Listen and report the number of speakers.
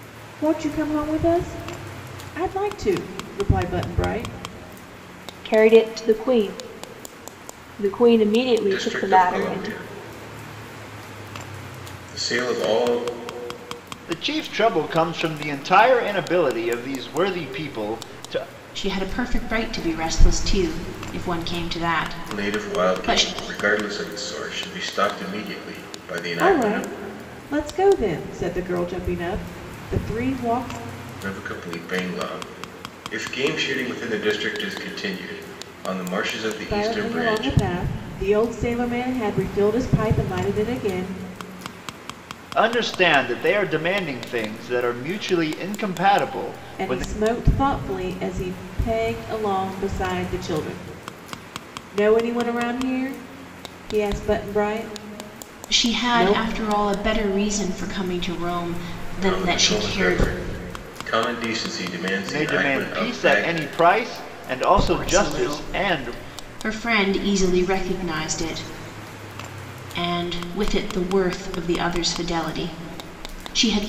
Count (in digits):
5